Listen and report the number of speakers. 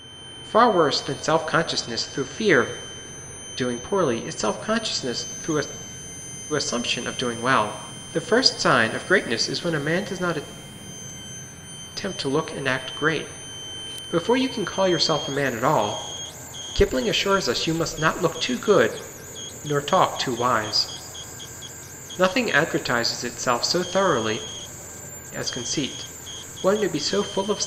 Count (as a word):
one